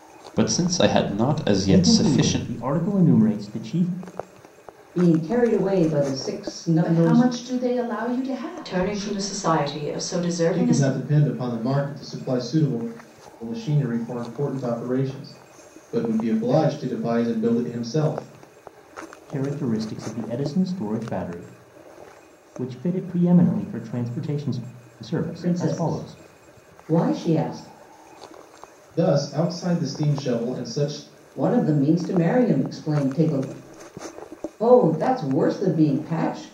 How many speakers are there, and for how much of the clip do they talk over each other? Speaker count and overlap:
6, about 9%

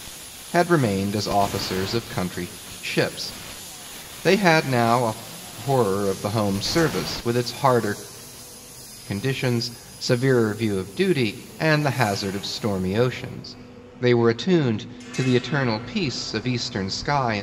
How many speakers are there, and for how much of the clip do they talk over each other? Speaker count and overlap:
1, no overlap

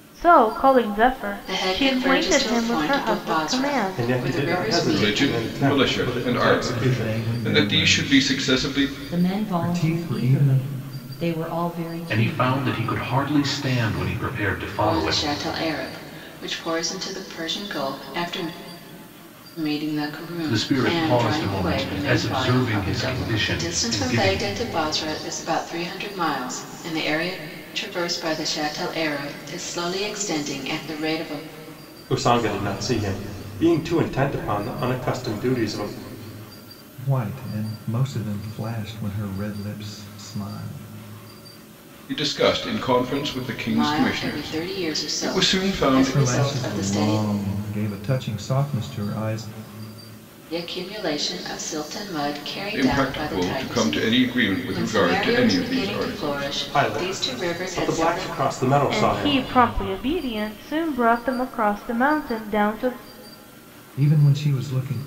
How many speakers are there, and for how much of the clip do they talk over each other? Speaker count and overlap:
7, about 36%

